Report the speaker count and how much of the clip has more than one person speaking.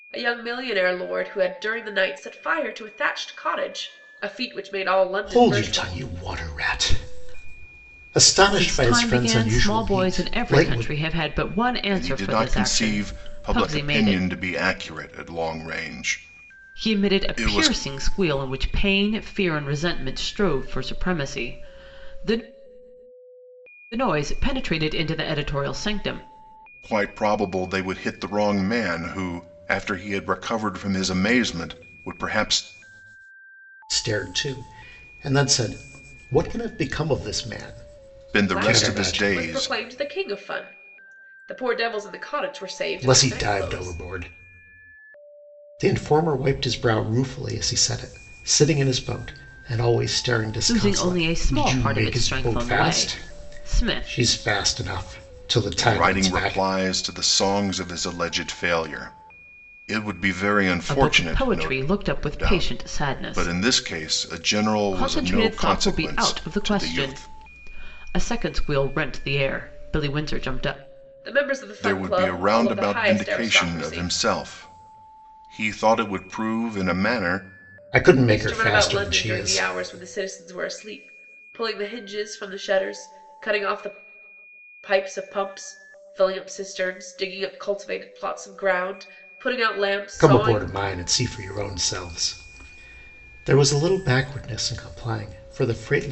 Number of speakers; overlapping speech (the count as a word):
four, about 23%